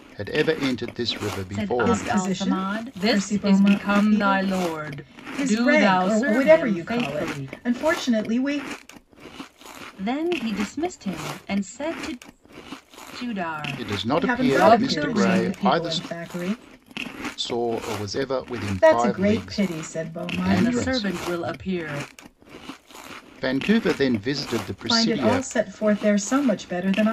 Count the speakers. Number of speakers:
3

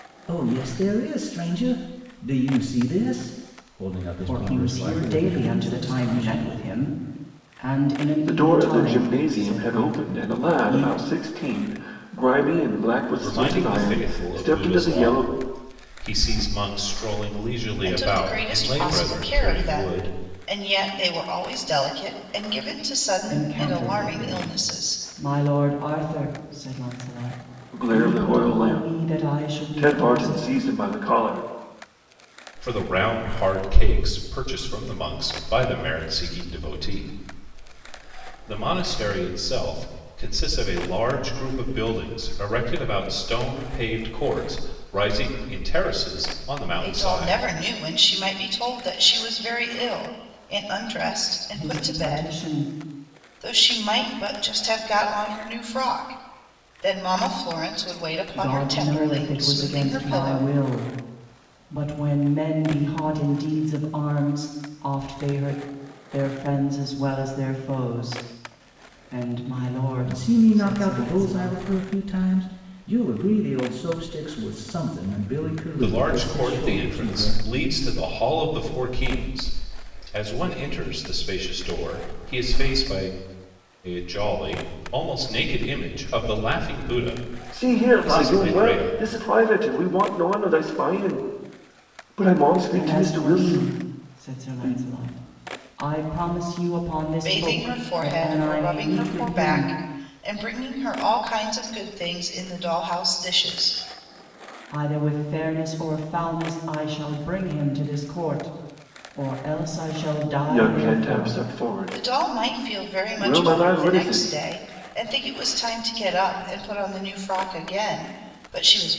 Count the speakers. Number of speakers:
5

